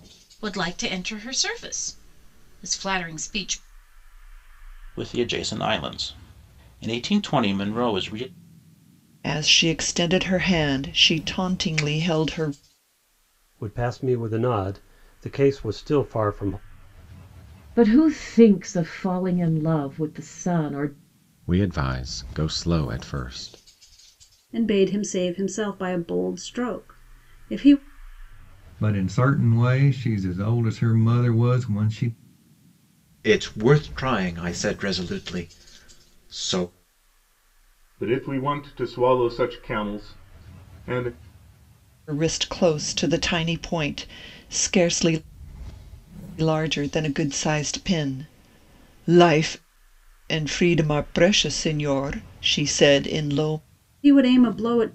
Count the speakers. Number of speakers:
ten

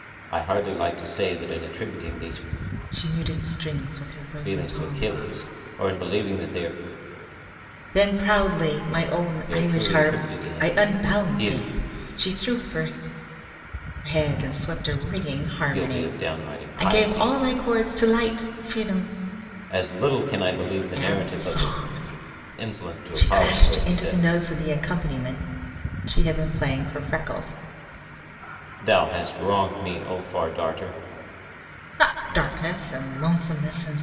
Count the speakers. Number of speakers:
two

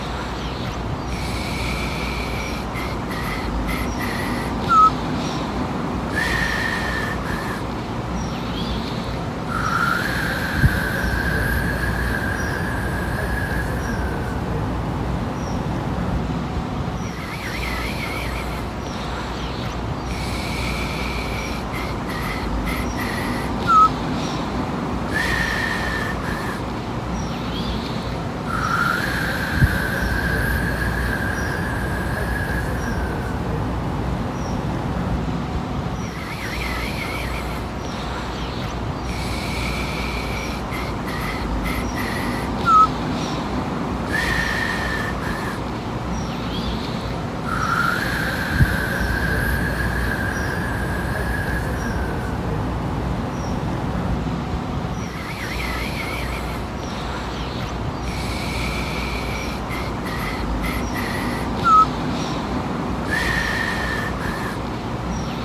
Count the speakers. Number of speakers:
zero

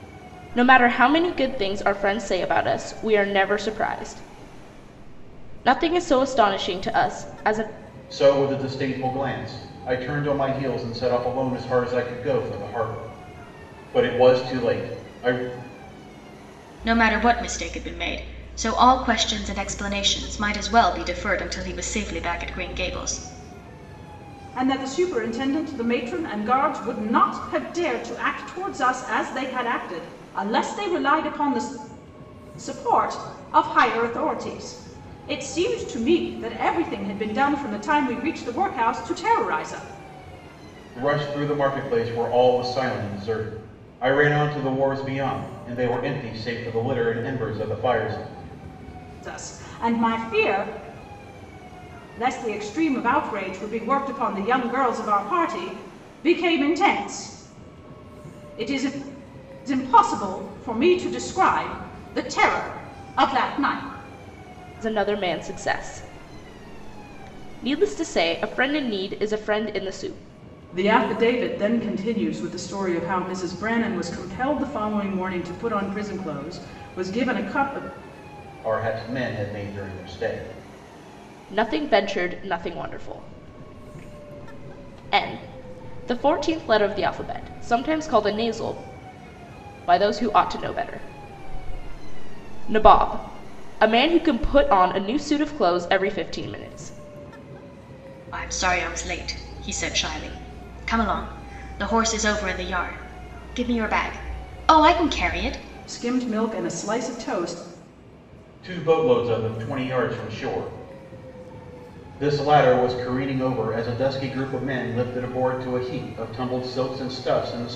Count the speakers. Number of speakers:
four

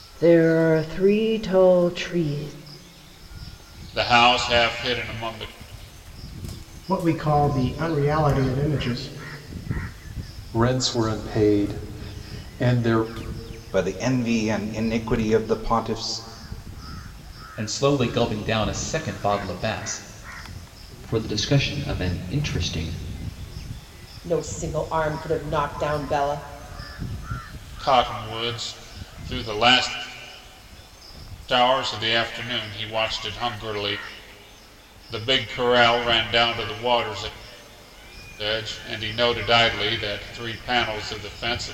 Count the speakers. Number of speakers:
eight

